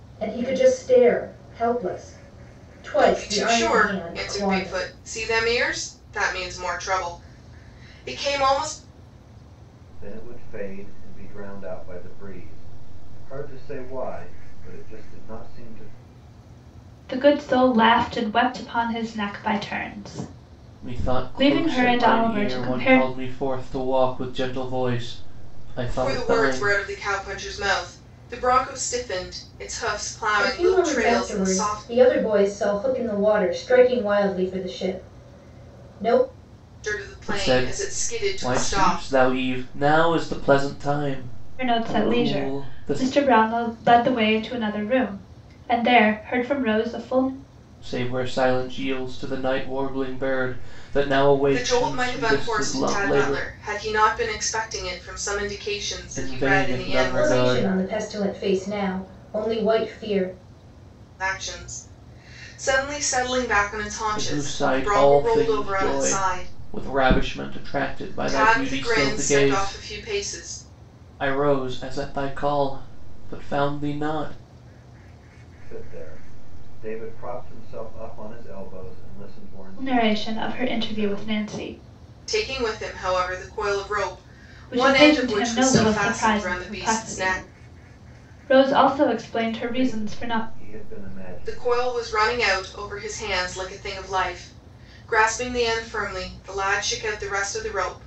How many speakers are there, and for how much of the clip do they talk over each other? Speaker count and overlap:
5, about 24%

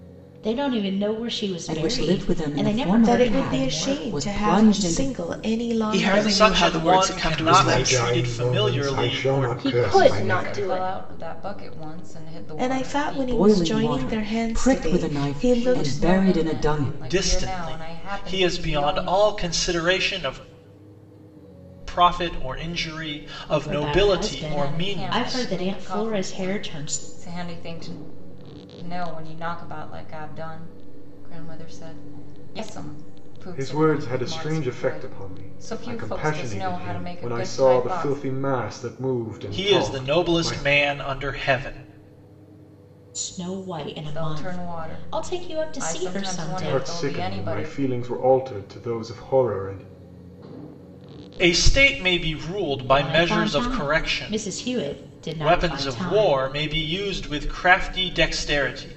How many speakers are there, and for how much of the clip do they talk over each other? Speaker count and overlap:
8, about 52%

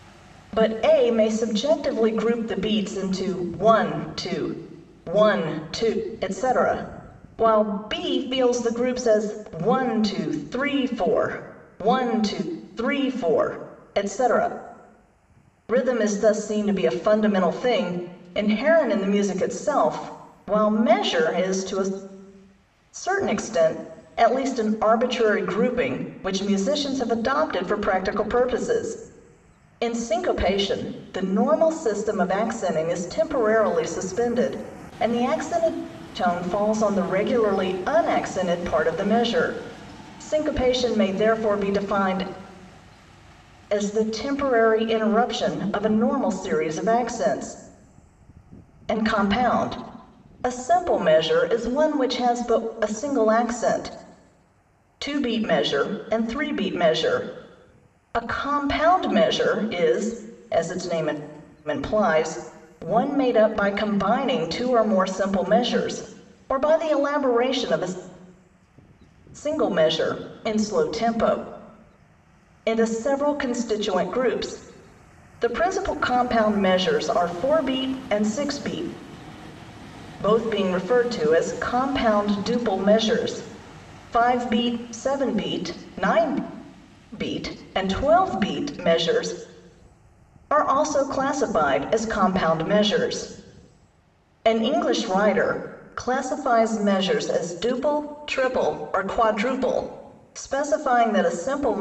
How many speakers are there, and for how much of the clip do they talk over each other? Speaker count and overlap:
1, no overlap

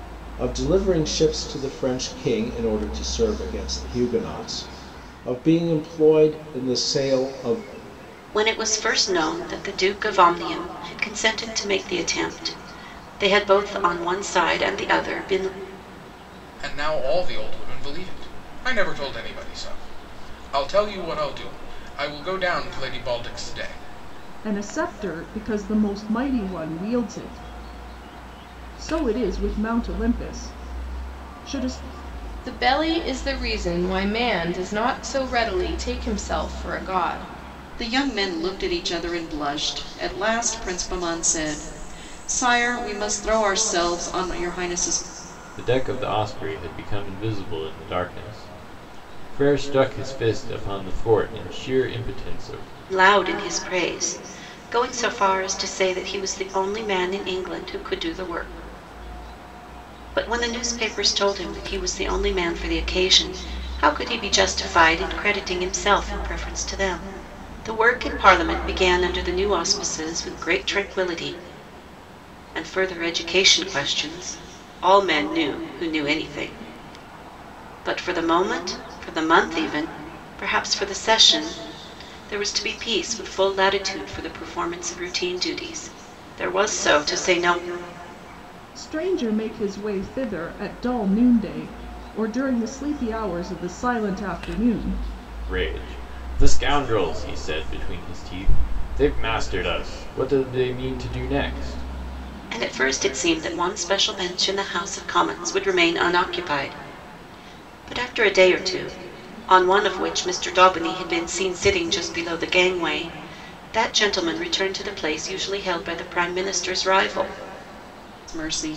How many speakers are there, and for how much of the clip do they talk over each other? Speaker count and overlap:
7, no overlap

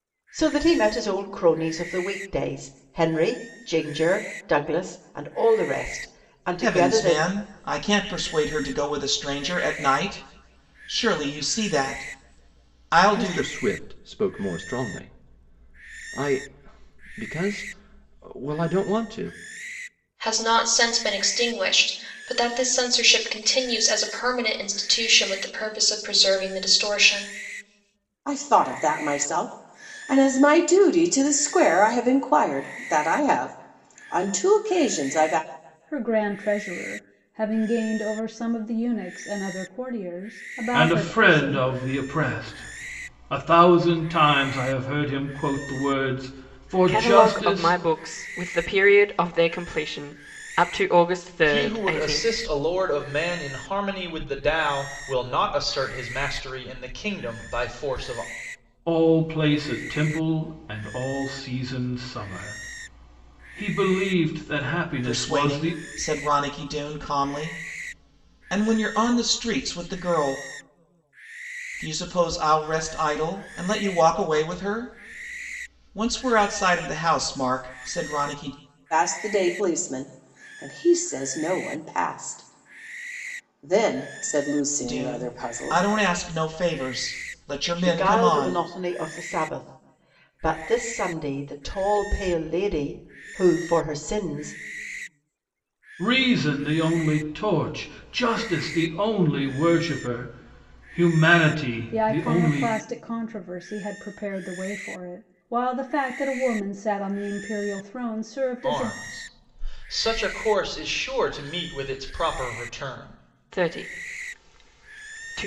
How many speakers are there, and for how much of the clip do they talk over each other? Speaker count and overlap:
9, about 7%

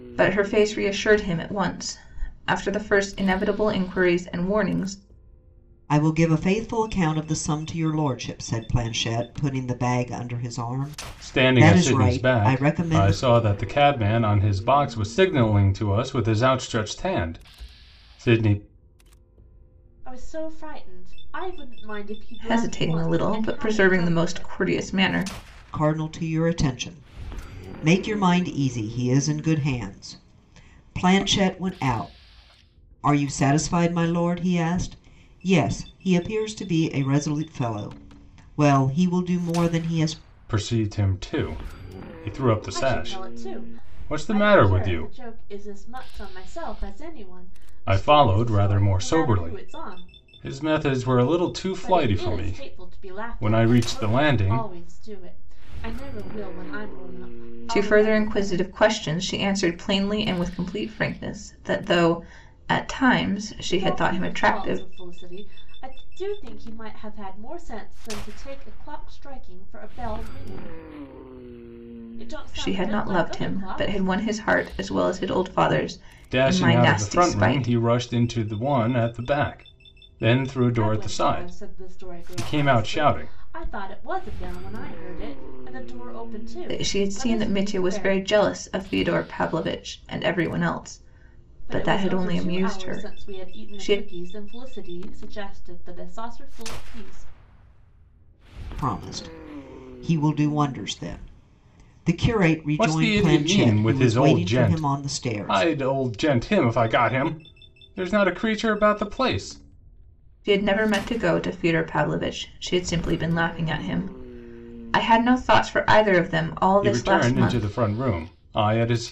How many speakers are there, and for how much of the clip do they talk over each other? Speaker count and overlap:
4, about 23%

